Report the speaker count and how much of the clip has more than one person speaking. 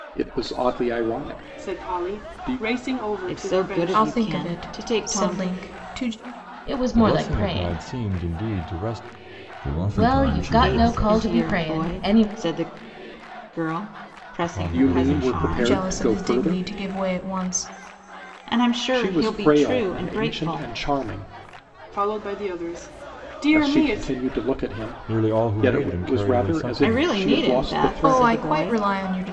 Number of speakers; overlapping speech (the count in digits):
7, about 51%